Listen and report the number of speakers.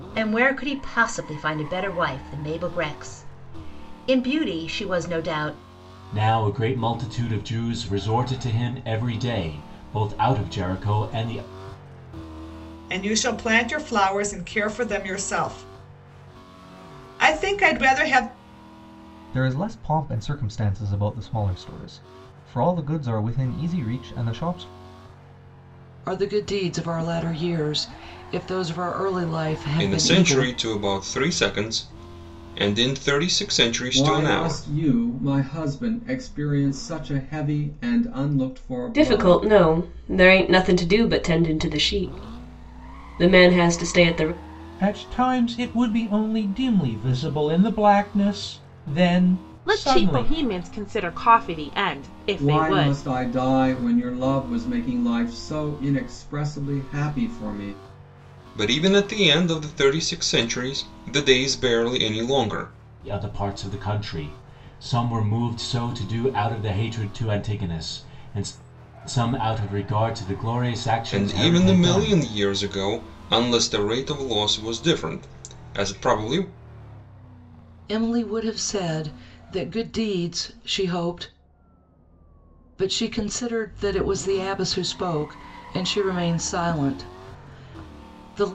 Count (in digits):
10